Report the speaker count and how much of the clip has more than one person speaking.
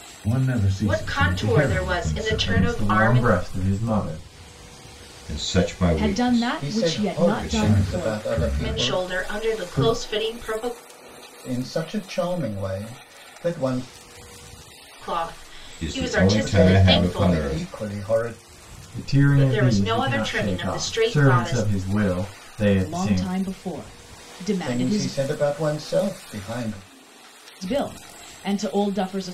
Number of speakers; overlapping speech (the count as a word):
six, about 41%